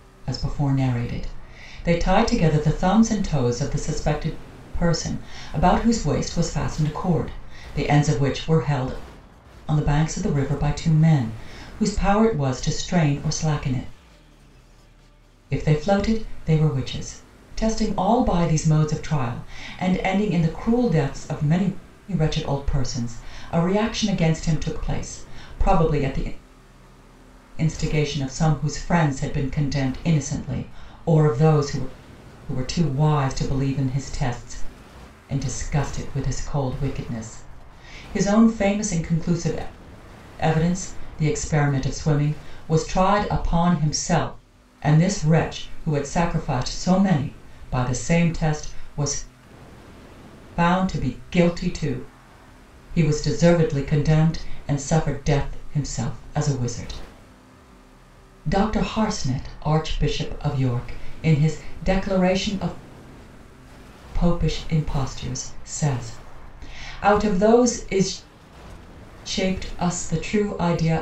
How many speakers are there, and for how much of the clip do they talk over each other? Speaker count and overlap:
1, no overlap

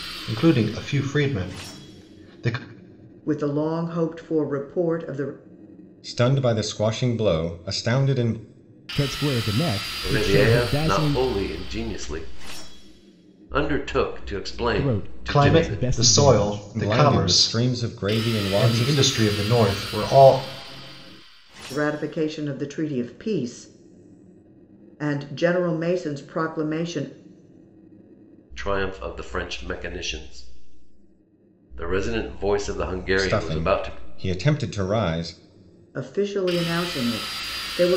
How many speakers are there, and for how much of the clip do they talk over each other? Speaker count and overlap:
5, about 14%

